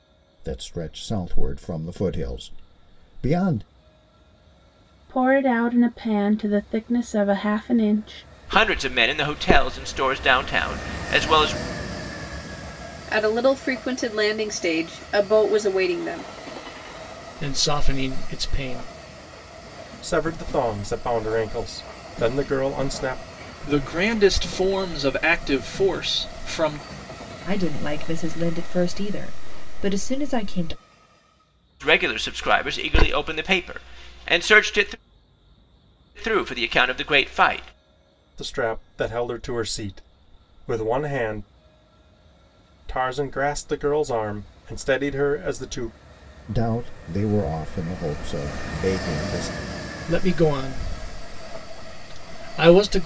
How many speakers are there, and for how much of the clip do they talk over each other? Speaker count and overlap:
8, no overlap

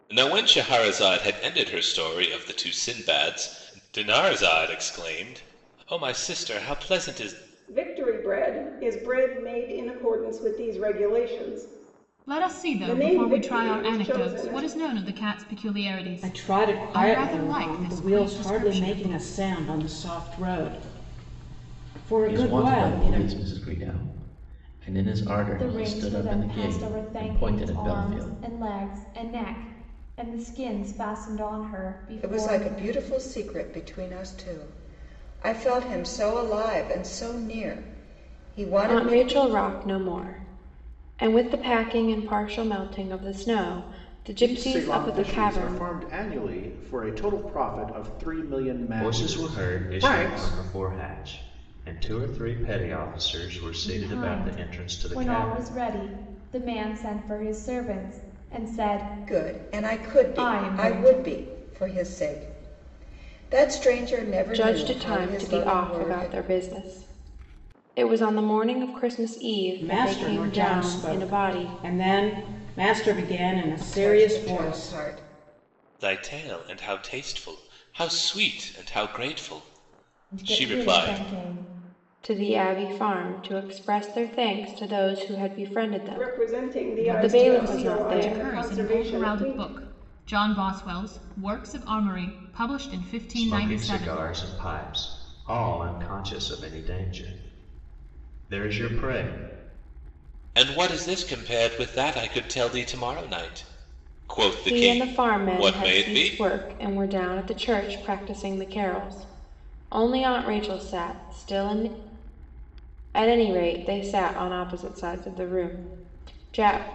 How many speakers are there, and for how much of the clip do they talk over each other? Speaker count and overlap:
10, about 26%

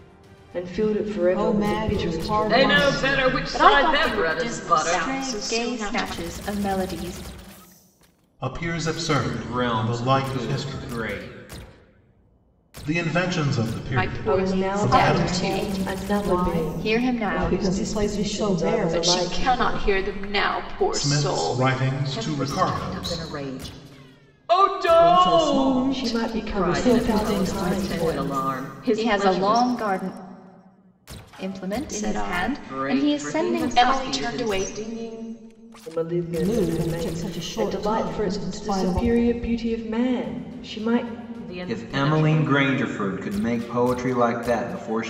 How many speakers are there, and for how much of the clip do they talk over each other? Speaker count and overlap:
7, about 57%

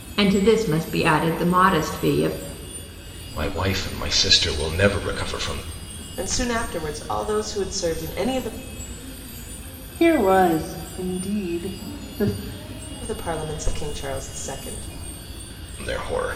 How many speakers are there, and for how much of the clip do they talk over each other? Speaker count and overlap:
4, no overlap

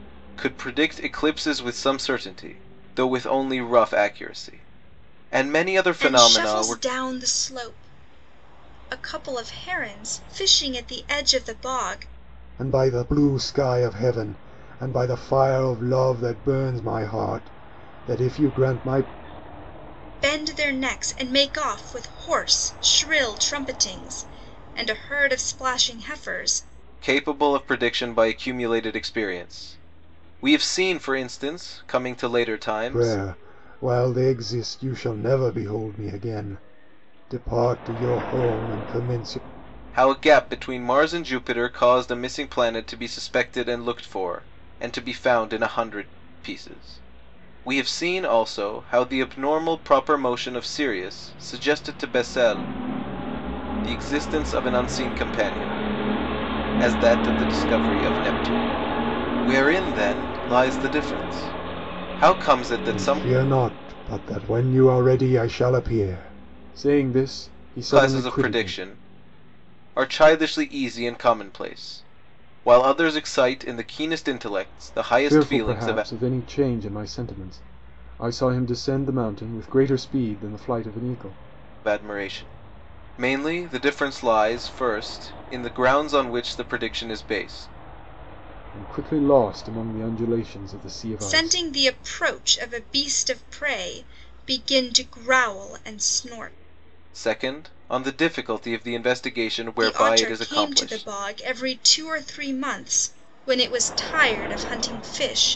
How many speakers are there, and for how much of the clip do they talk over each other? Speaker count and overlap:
3, about 5%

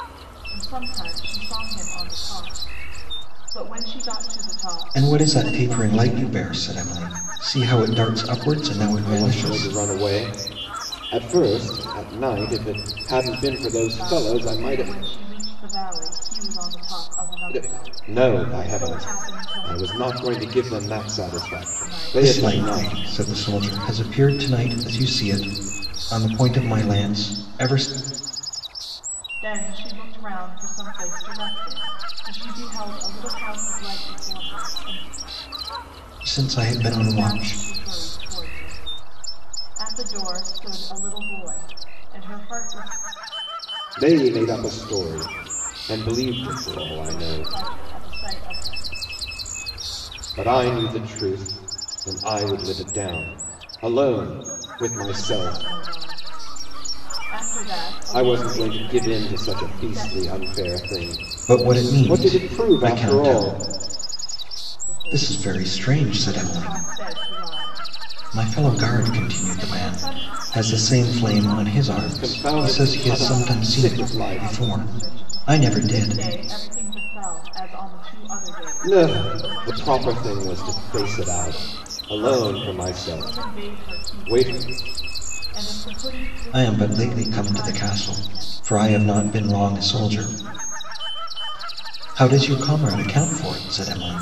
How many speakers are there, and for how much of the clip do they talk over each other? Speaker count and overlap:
3, about 29%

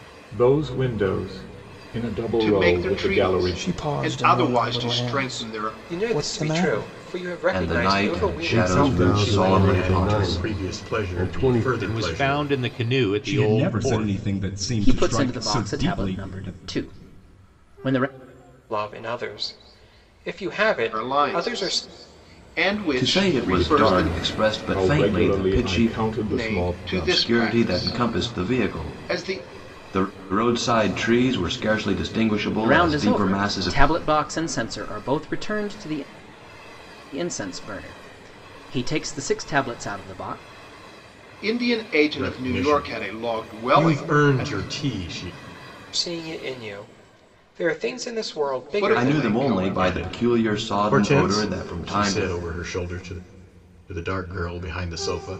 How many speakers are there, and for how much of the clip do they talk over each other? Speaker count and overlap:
10, about 49%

